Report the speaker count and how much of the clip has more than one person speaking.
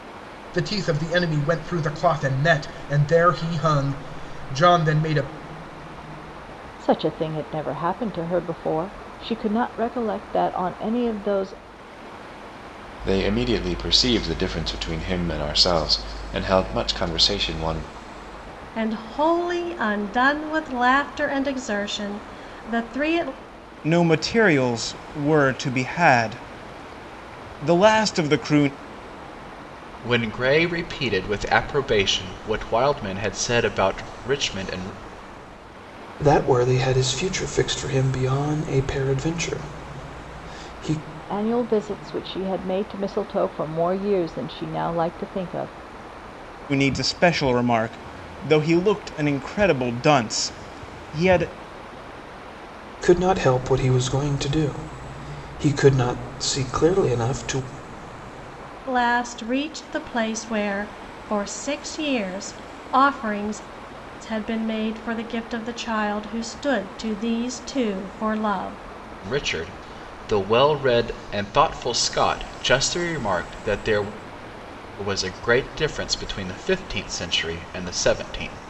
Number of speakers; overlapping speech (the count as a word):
seven, no overlap